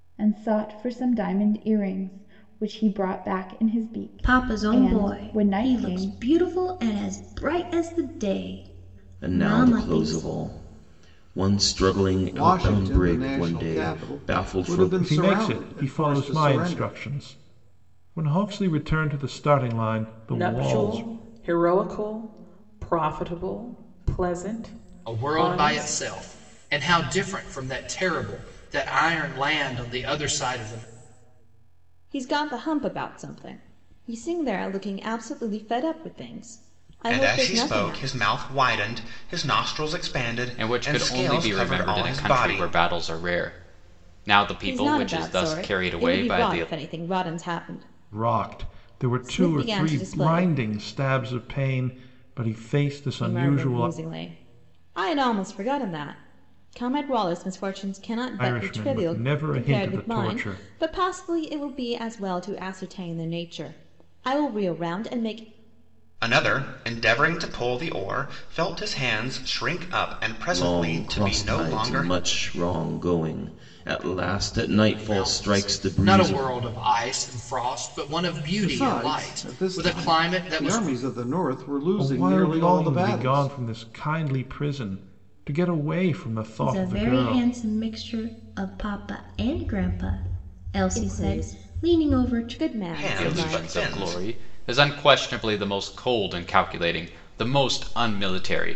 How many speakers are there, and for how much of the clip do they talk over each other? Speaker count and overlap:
10, about 31%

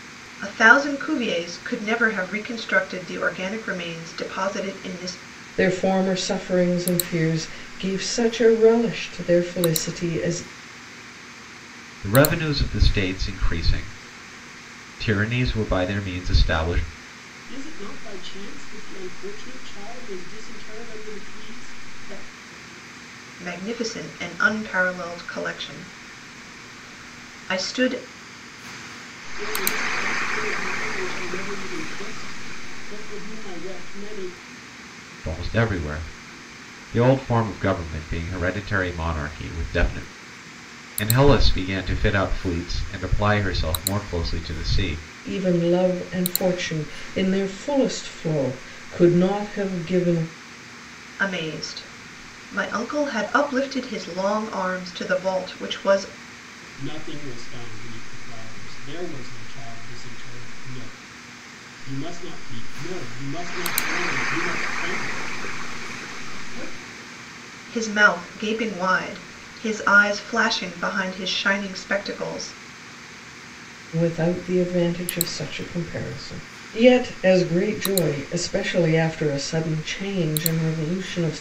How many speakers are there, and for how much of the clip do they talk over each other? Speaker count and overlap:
4, no overlap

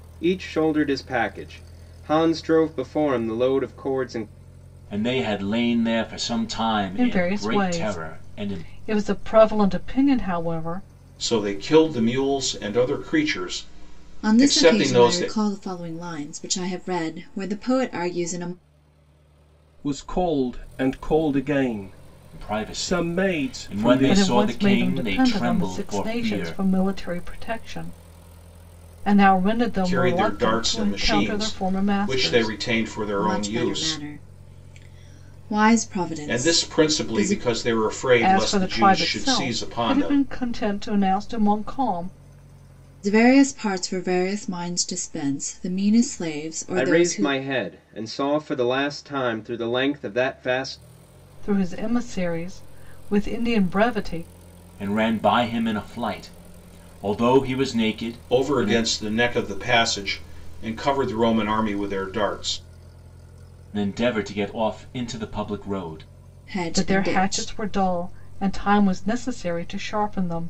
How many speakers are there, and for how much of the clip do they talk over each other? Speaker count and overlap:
6, about 23%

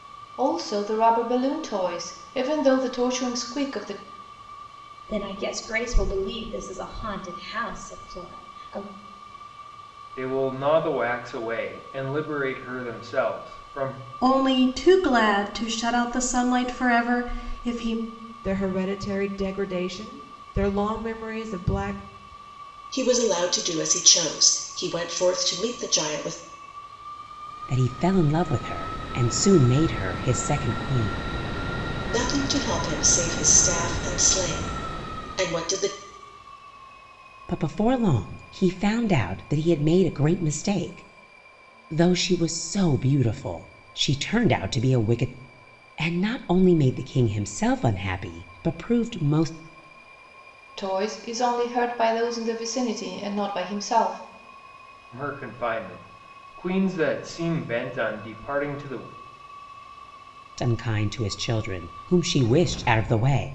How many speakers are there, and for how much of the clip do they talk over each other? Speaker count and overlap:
7, no overlap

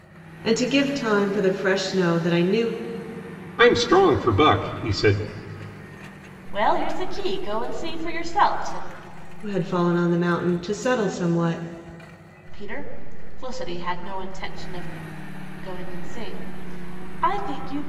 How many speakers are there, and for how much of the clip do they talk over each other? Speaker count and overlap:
3, no overlap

